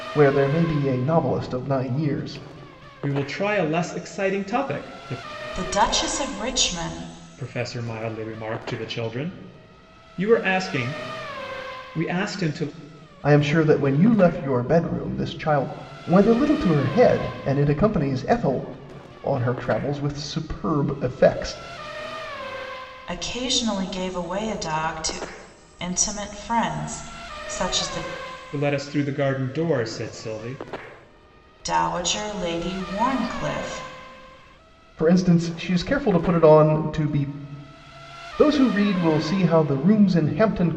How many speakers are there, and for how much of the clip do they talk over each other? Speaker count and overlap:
3, no overlap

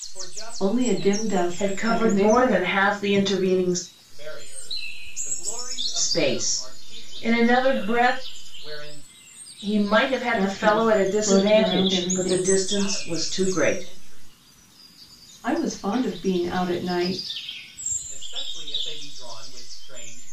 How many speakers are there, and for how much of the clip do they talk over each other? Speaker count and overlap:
3, about 40%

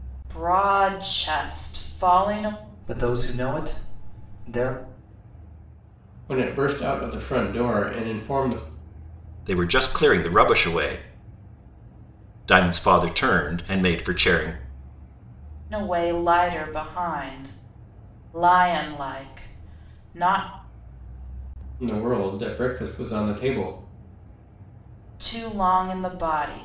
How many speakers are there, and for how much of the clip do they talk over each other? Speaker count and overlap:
4, no overlap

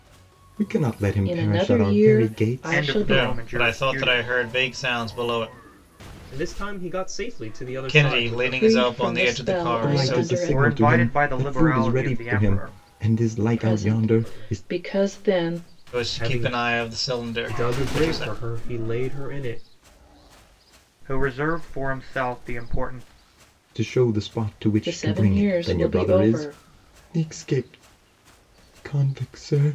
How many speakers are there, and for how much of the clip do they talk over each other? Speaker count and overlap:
5, about 45%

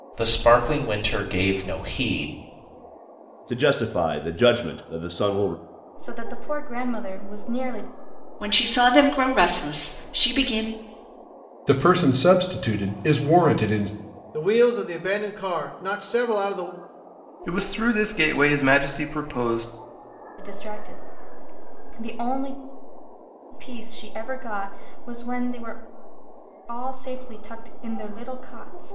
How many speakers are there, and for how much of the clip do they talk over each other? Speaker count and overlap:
7, no overlap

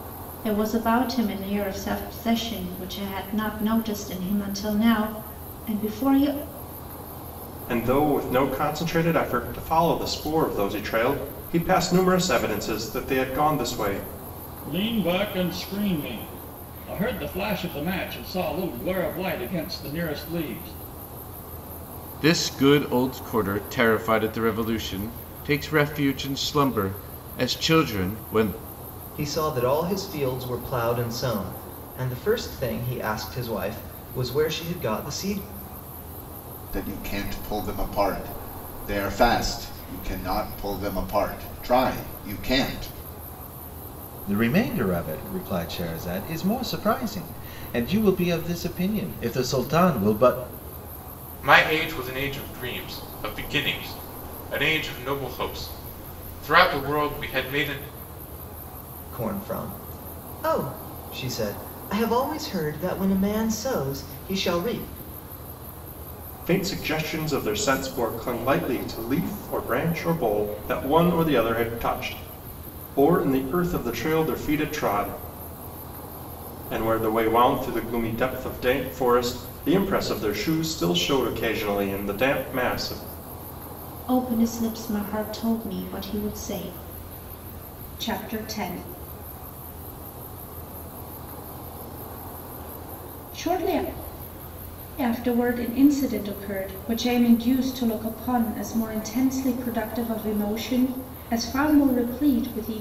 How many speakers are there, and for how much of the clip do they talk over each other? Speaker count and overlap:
8, no overlap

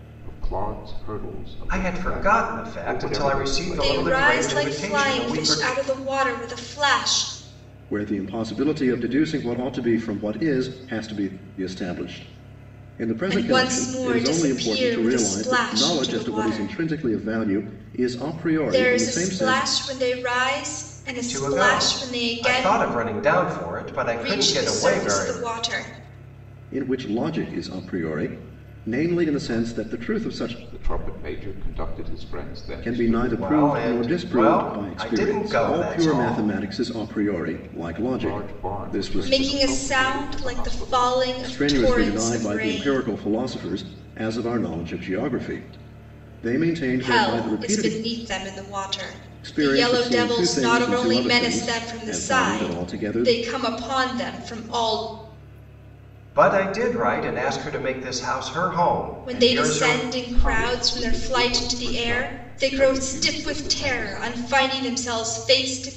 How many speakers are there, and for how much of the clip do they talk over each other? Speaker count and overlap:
4, about 47%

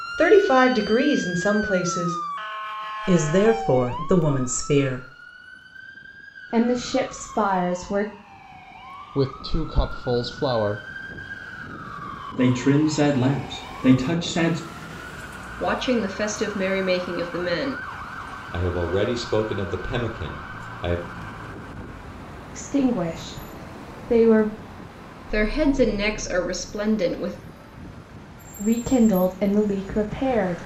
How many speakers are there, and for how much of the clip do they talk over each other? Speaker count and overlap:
7, no overlap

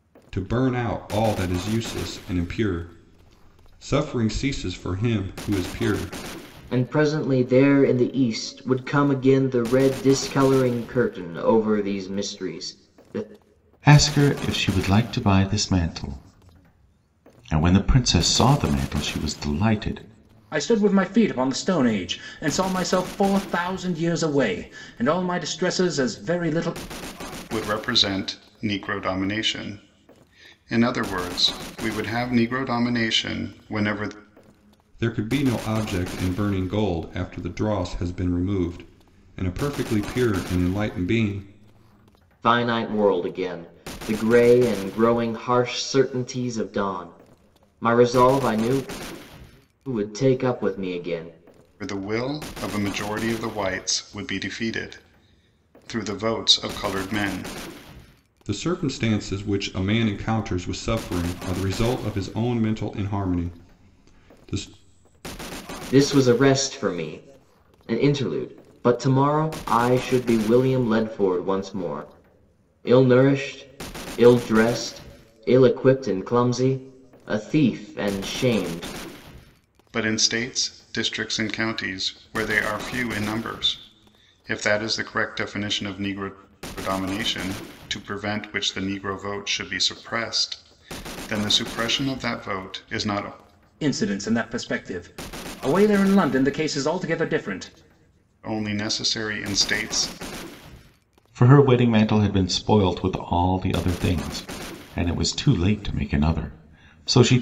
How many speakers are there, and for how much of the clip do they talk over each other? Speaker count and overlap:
5, no overlap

